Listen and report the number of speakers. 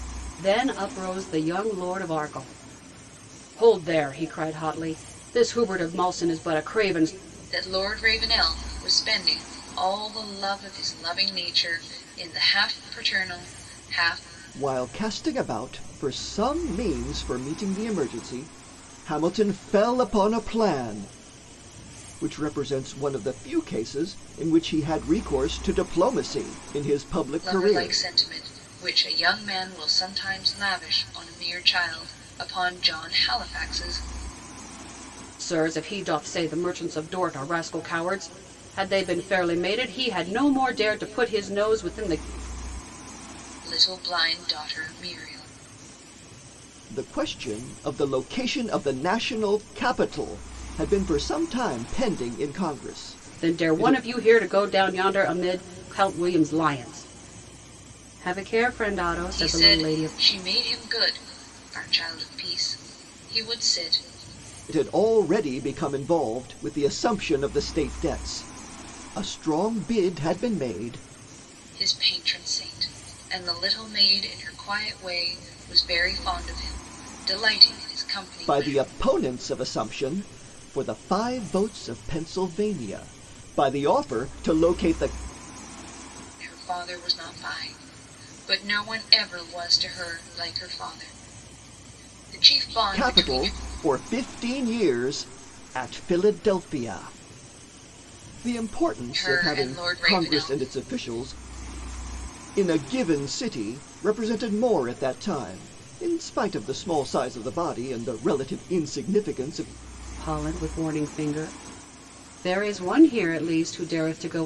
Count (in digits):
3